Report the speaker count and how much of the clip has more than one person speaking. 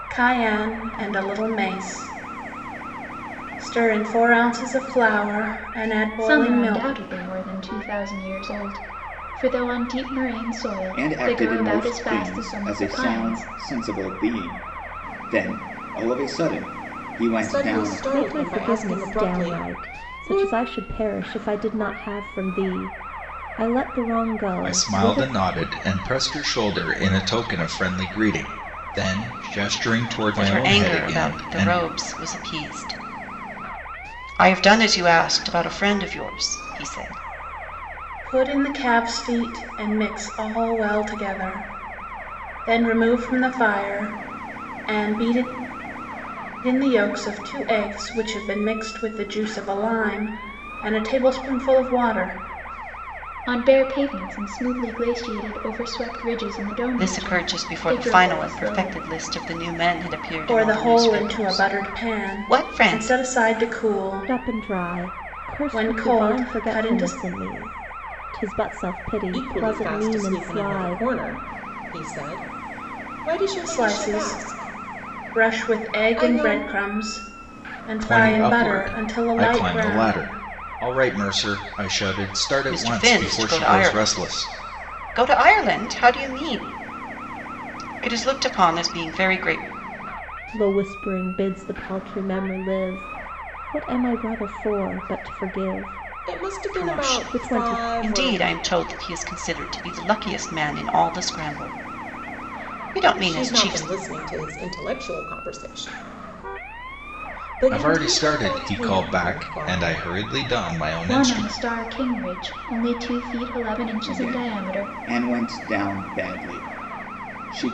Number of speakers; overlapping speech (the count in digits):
7, about 27%